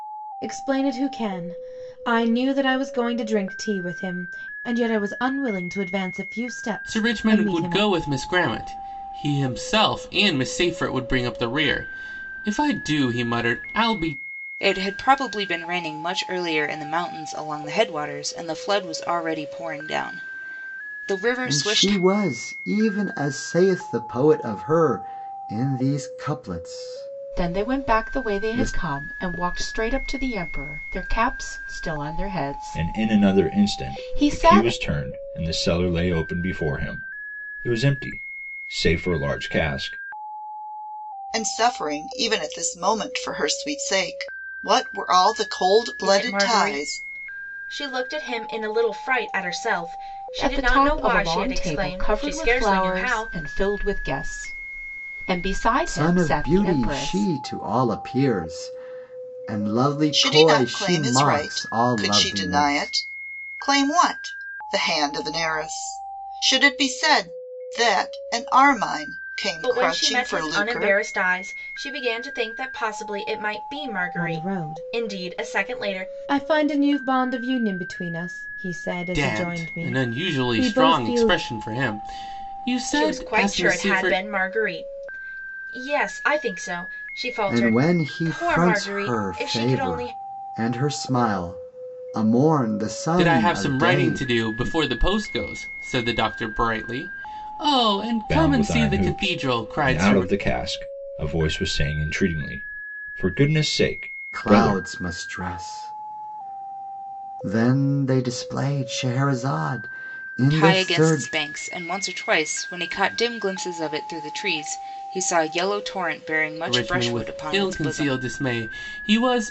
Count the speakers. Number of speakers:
8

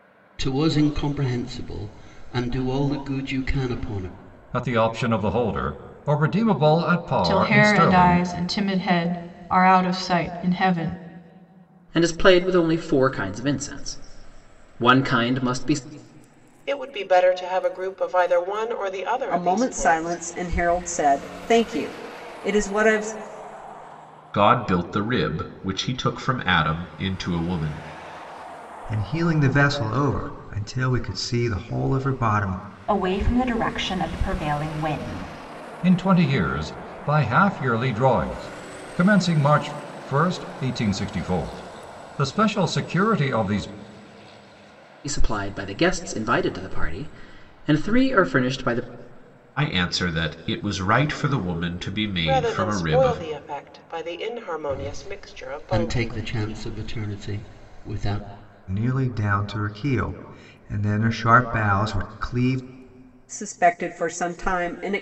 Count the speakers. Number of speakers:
9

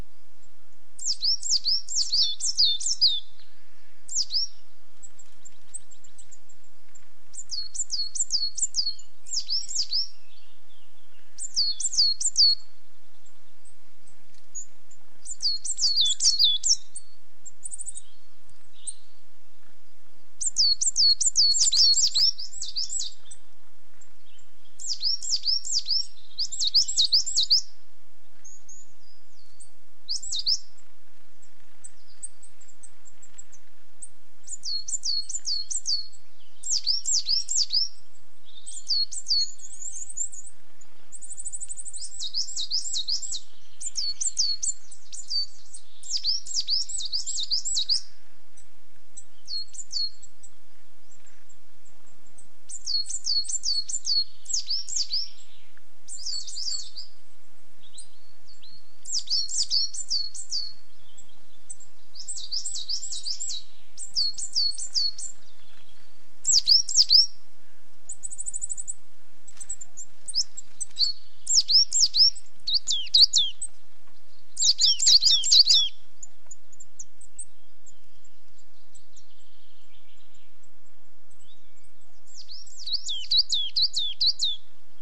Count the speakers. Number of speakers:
0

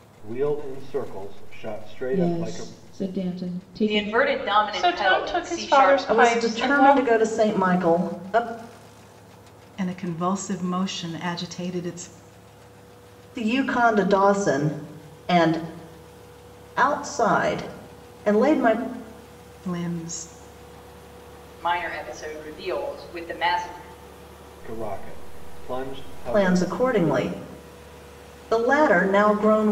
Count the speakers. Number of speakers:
6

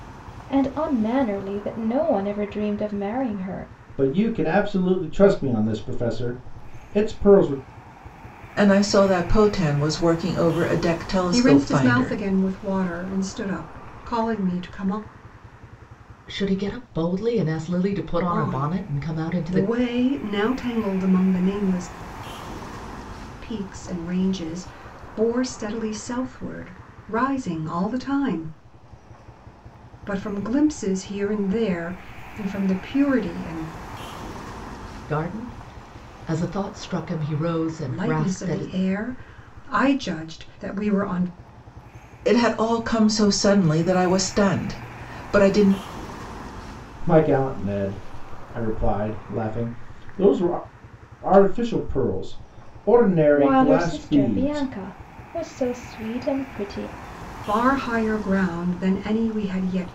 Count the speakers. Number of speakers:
5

